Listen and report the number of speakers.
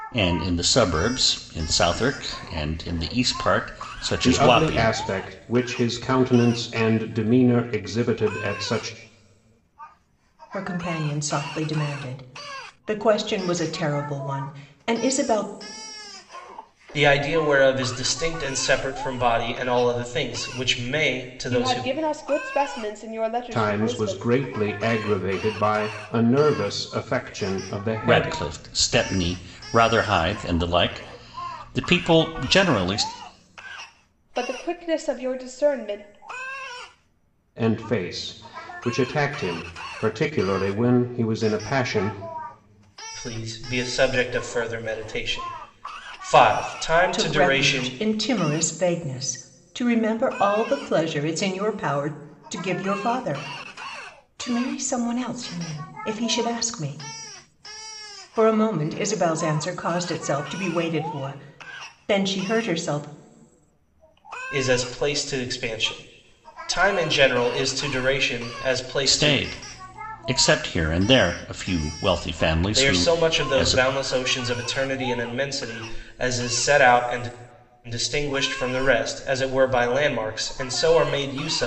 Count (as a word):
five